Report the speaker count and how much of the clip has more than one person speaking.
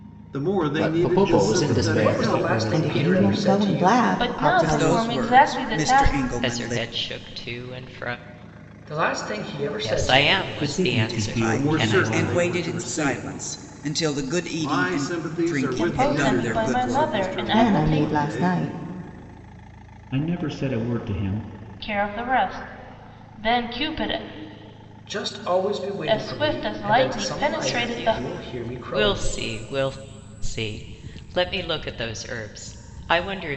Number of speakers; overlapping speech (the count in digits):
8, about 49%